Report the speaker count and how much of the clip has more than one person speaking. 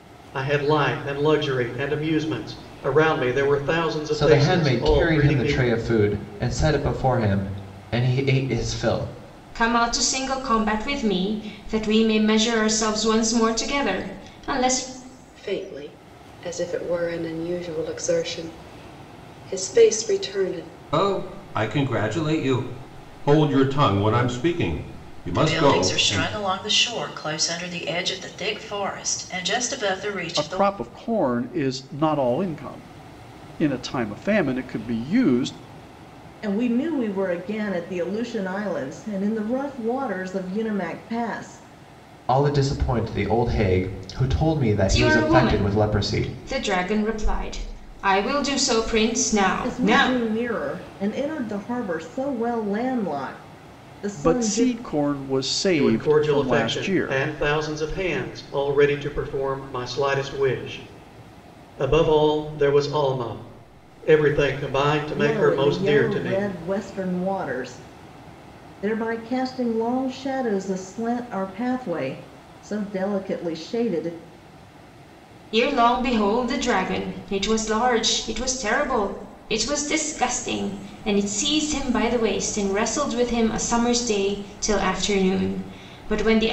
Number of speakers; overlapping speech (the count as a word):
eight, about 10%